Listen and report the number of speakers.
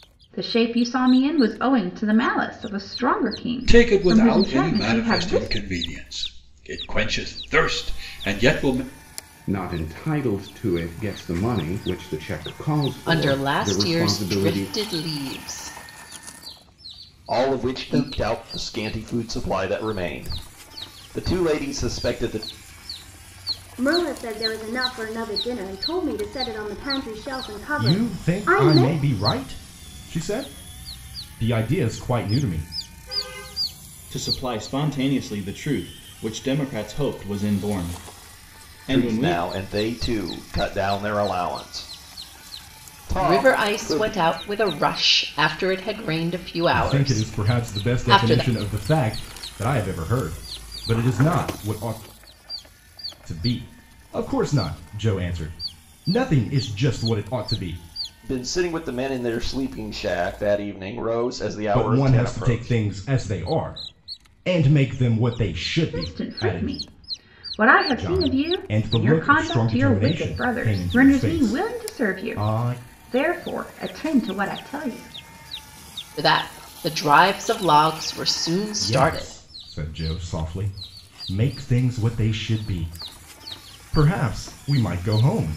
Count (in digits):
8